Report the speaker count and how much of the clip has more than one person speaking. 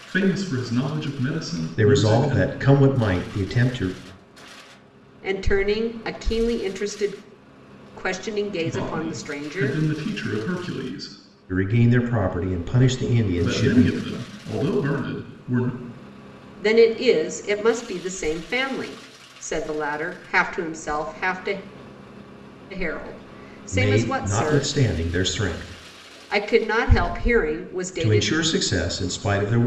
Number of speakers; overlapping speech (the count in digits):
3, about 13%